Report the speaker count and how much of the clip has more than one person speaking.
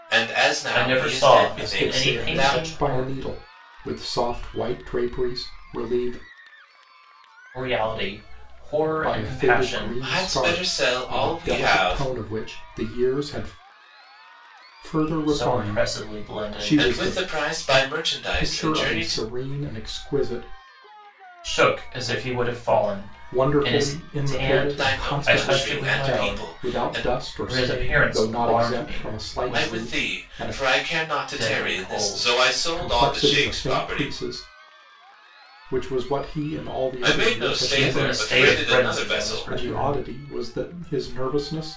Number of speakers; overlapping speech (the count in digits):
3, about 50%